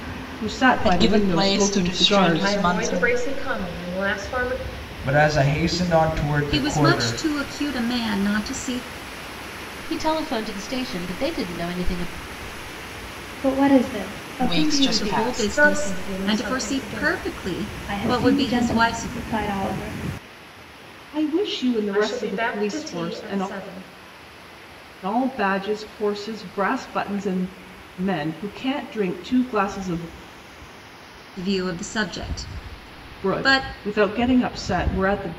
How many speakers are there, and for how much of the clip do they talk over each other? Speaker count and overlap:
7, about 26%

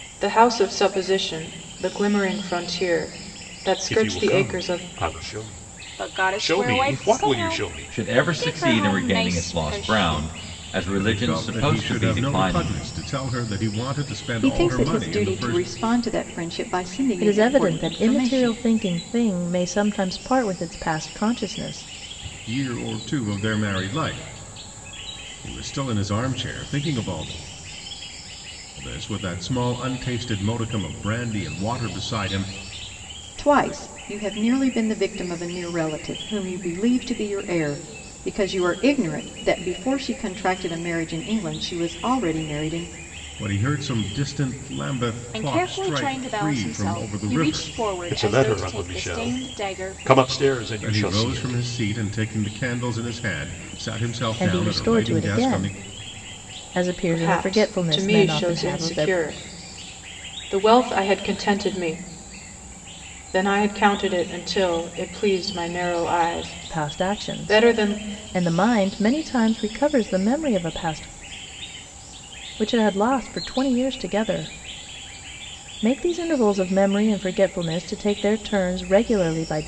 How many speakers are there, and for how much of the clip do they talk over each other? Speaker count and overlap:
7, about 26%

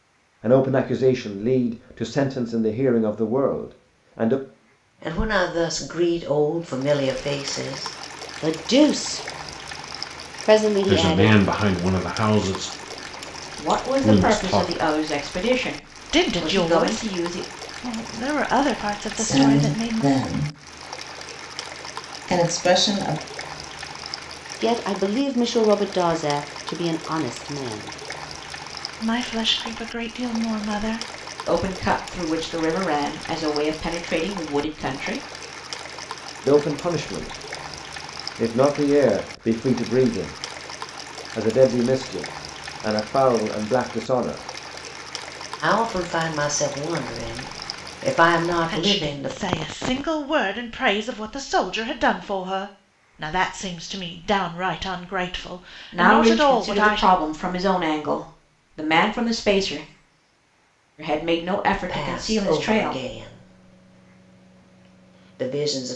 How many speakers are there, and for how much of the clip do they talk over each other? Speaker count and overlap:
7, about 11%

